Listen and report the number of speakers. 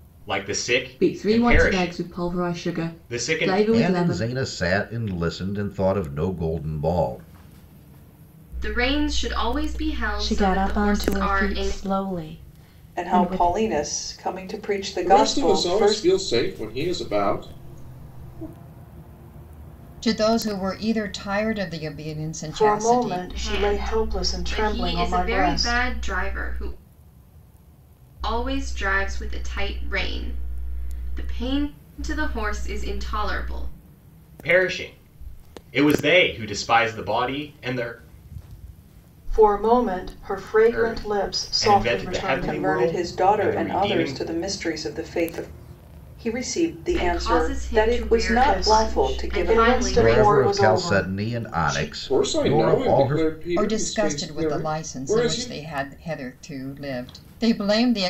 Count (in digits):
9